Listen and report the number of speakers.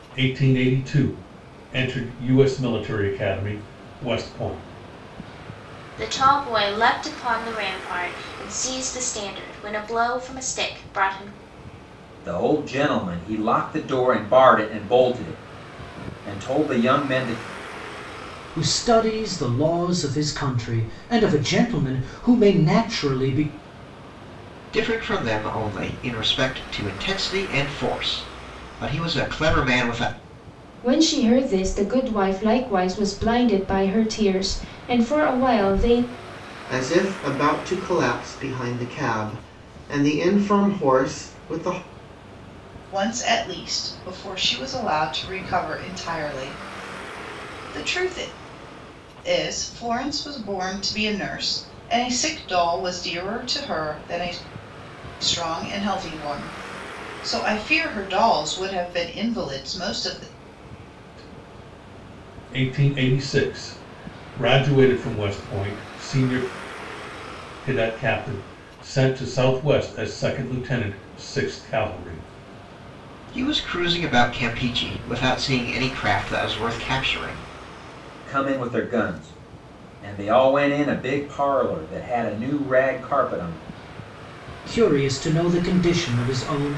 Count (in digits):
8